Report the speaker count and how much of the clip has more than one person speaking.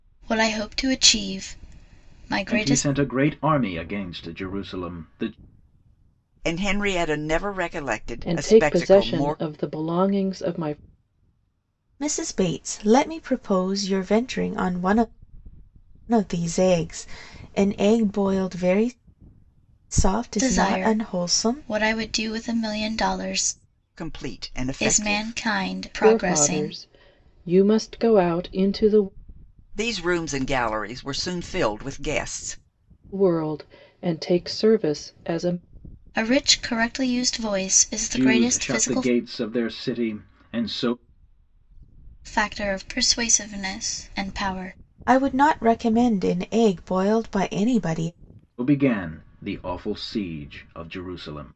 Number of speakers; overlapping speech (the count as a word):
five, about 11%